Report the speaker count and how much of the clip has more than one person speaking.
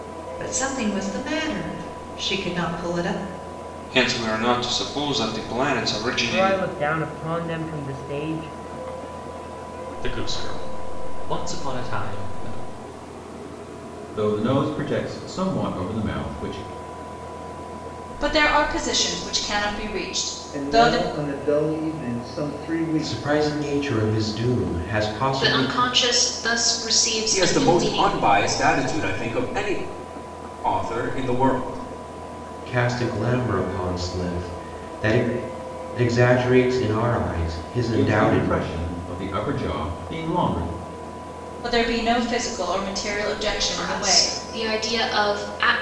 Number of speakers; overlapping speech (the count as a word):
ten, about 9%